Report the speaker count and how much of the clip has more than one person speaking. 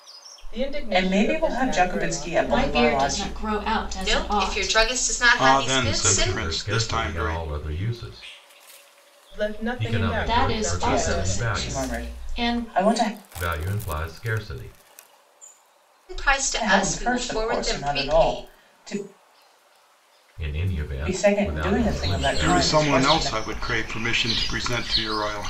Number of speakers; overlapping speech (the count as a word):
six, about 49%